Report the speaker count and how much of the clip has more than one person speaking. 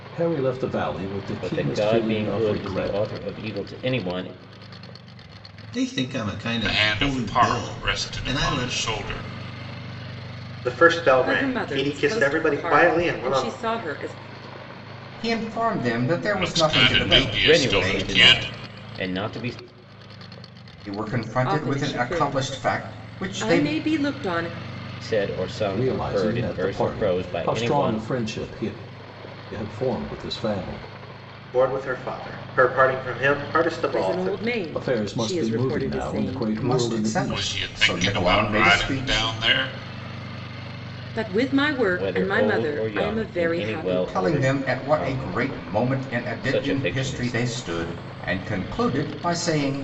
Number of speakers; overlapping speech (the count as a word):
seven, about 47%